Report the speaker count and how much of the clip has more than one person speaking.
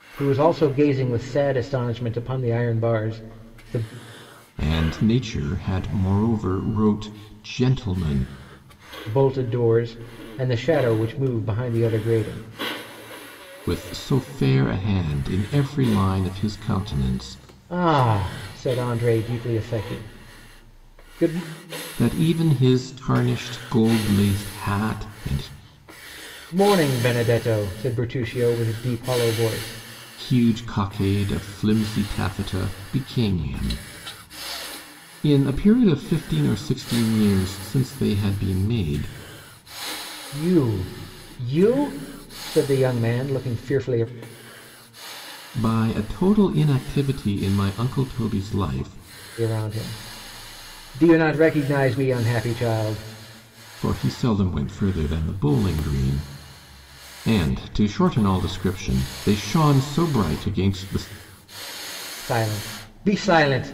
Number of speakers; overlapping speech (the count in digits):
2, no overlap